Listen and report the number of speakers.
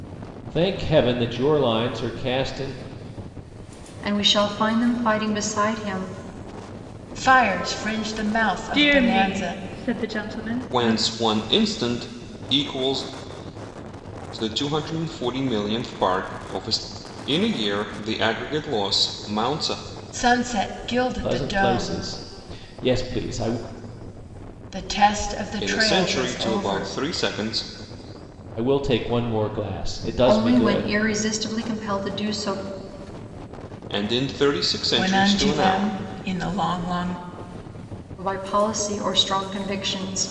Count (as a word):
five